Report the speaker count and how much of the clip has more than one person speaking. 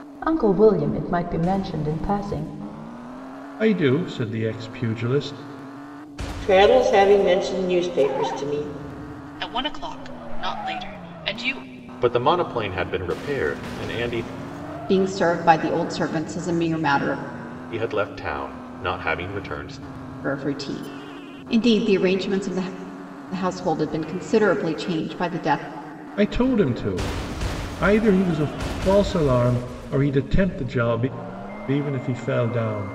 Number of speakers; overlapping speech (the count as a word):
six, no overlap